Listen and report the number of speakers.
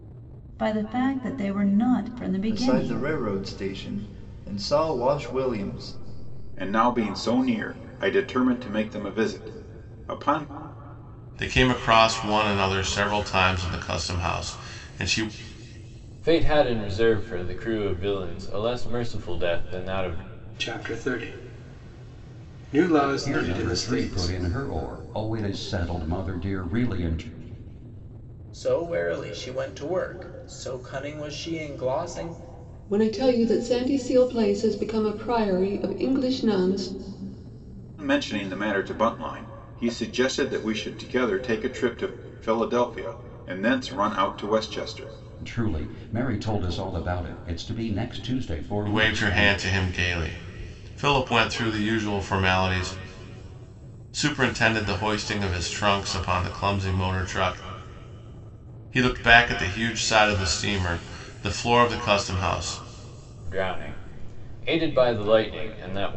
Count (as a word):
nine